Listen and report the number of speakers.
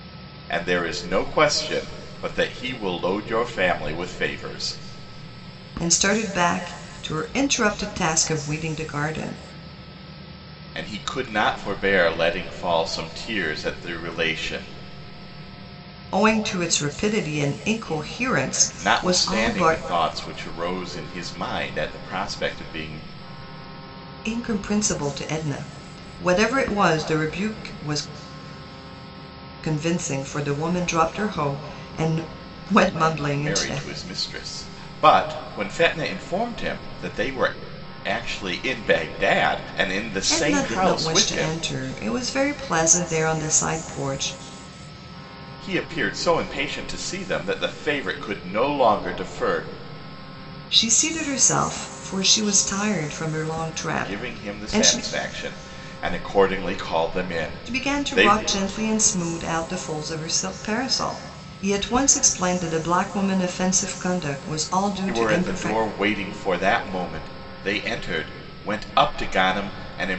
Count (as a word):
two